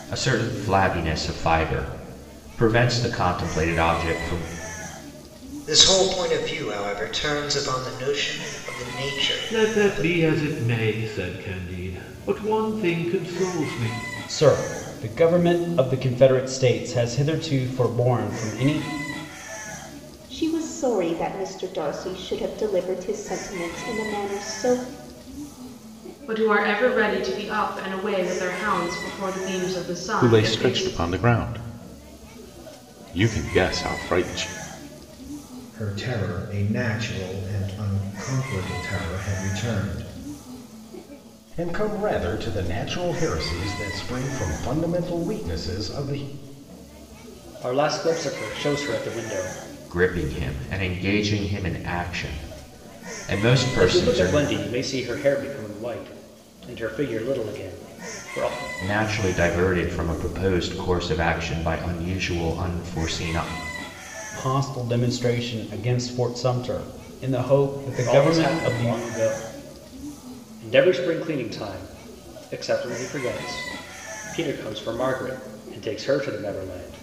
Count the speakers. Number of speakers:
10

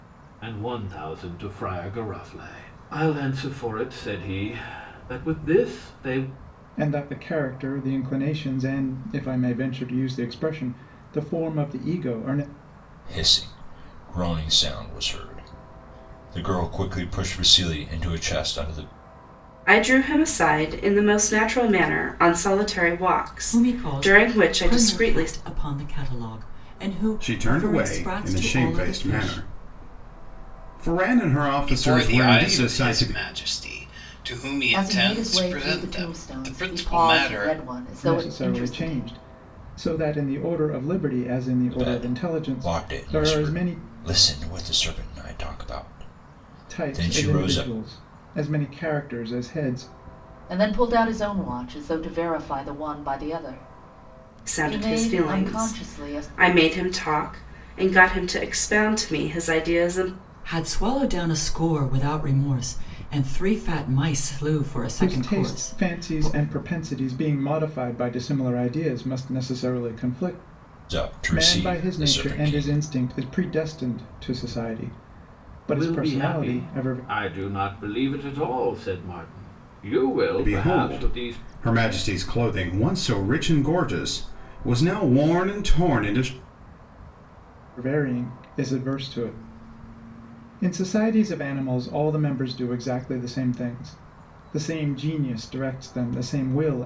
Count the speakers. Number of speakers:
8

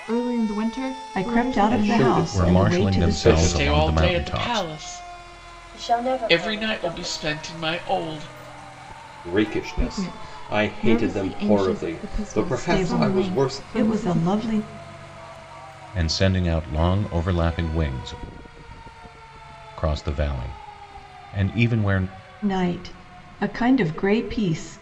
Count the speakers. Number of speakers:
6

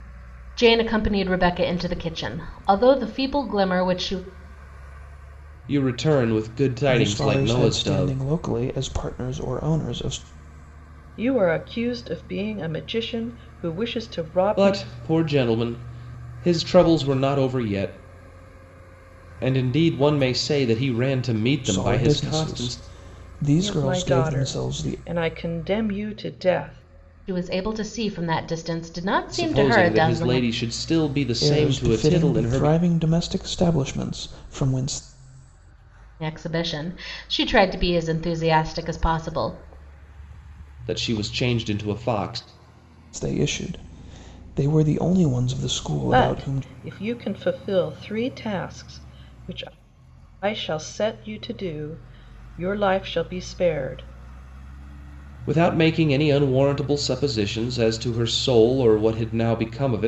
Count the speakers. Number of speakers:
4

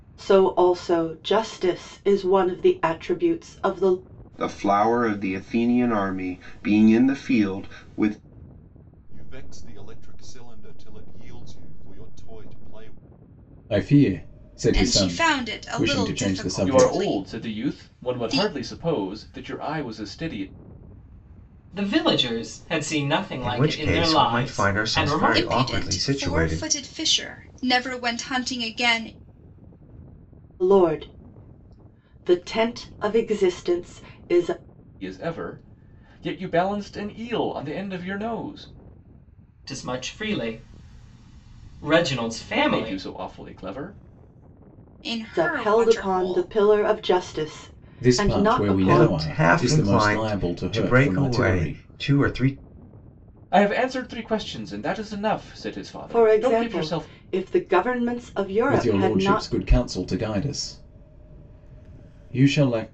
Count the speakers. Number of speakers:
8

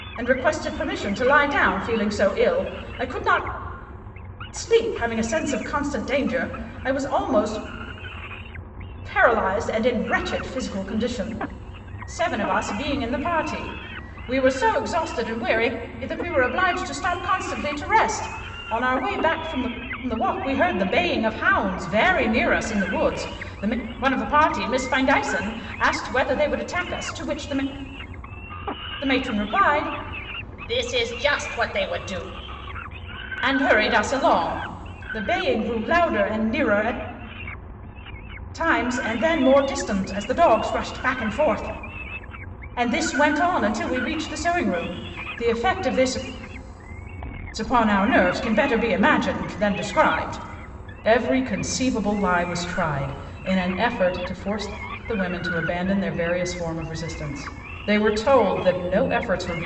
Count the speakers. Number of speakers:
1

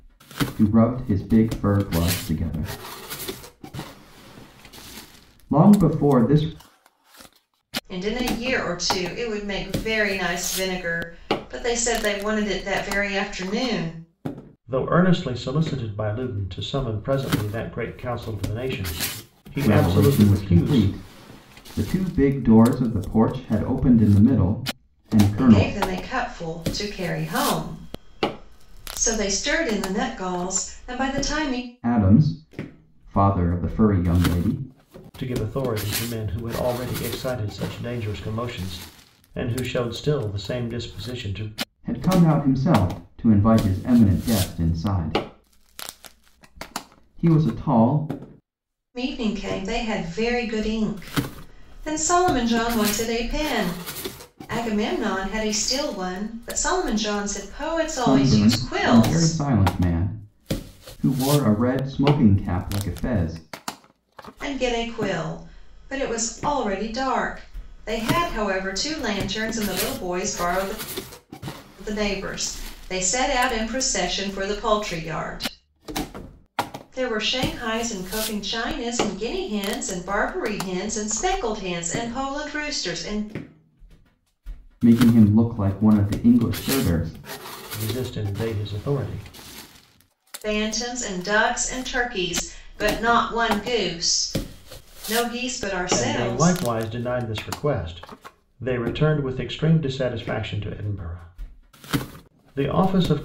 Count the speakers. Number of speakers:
3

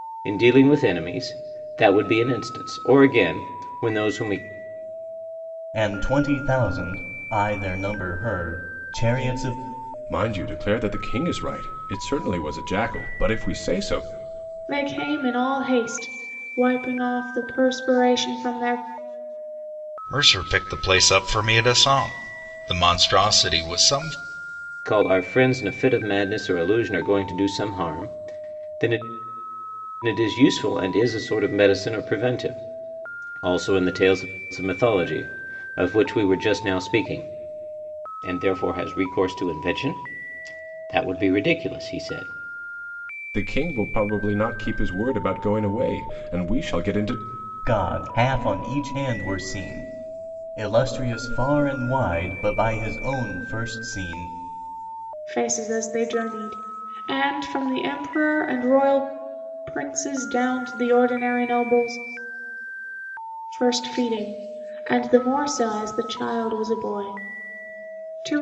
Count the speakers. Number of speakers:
5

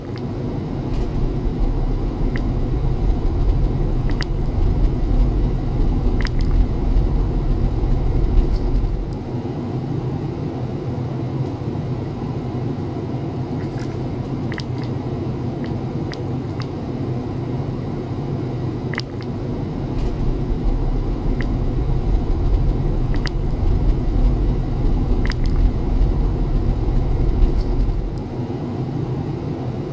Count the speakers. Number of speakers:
0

